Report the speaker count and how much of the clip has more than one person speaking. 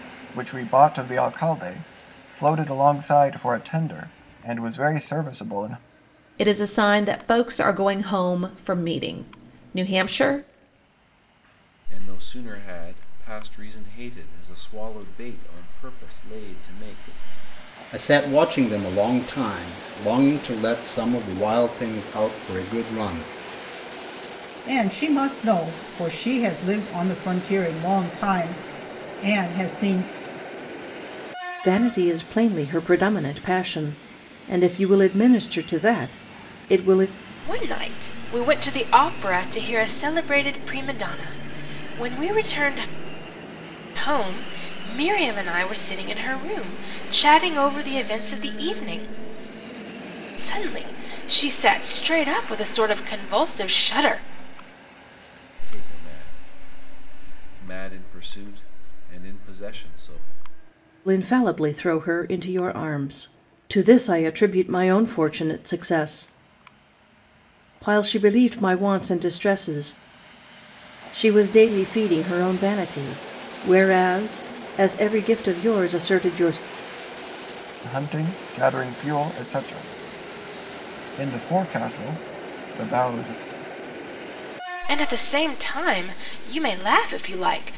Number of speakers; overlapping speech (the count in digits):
7, no overlap